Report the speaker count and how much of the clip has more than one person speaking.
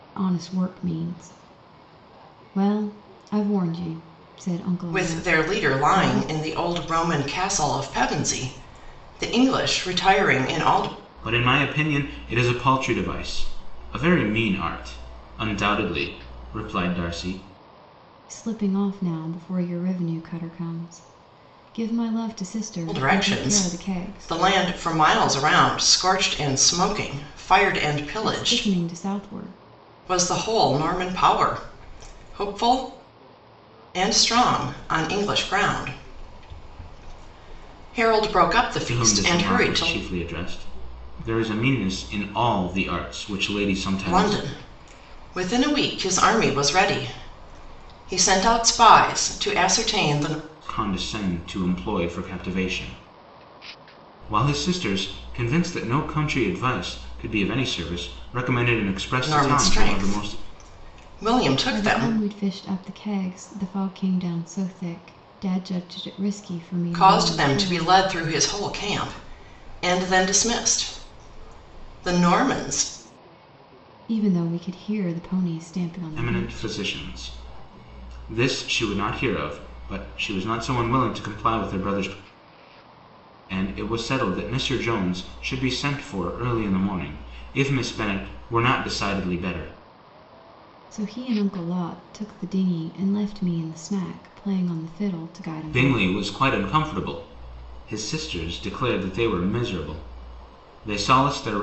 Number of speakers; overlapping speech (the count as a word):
three, about 9%